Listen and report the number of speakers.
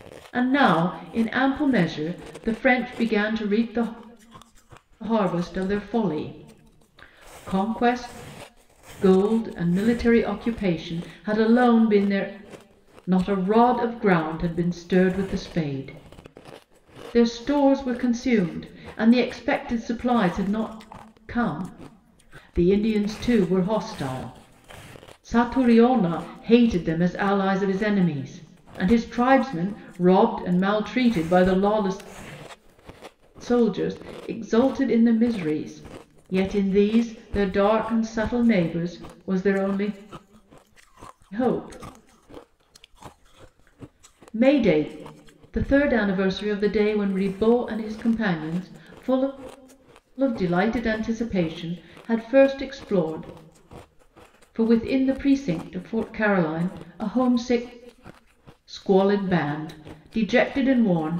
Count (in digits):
1